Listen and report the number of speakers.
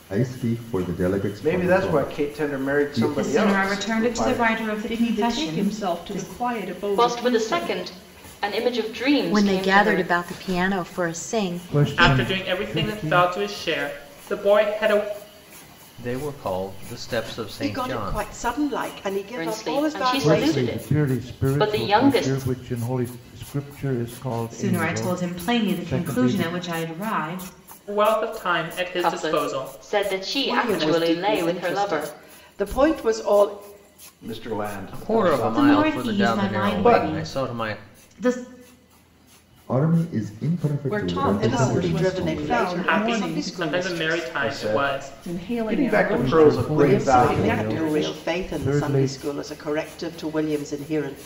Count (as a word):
ten